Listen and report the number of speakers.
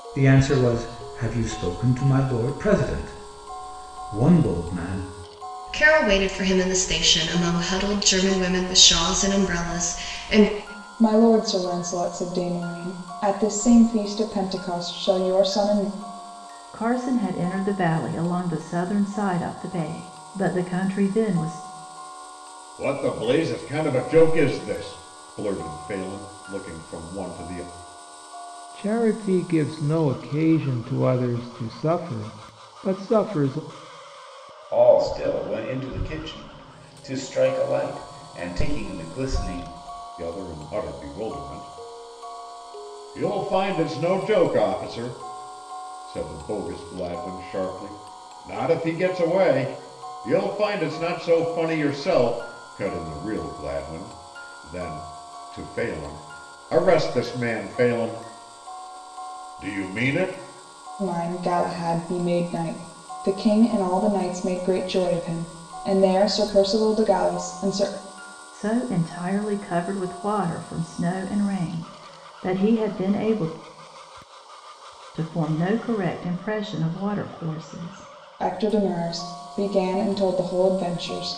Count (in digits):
7